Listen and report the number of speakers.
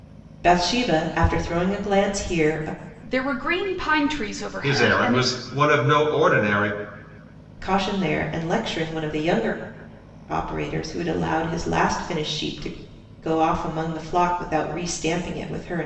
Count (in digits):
3